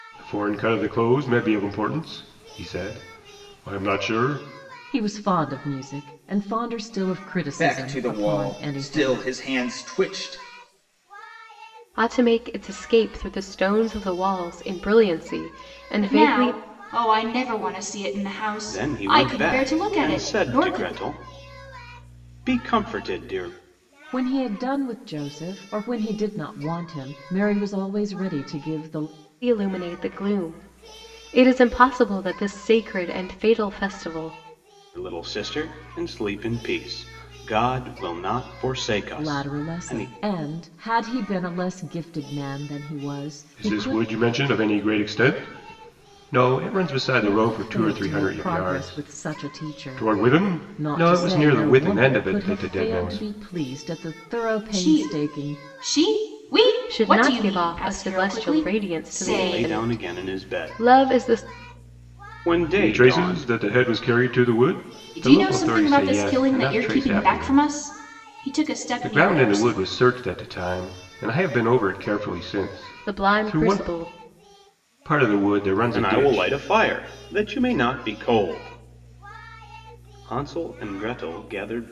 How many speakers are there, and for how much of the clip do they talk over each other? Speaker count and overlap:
6, about 28%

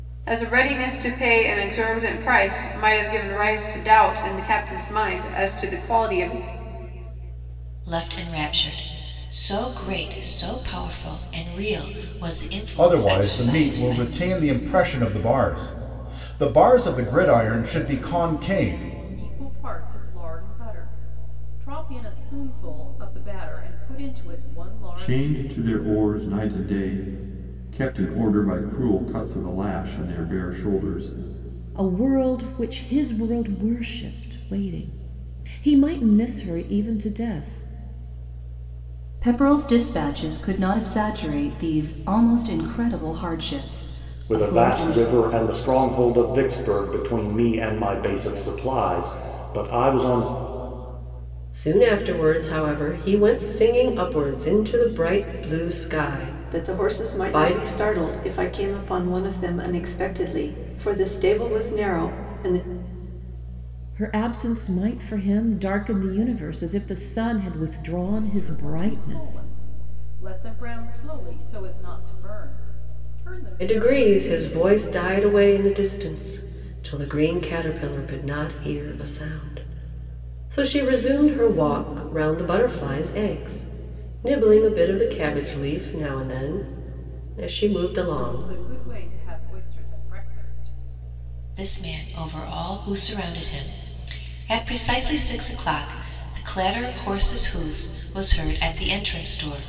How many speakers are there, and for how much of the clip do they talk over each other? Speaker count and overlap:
10, about 6%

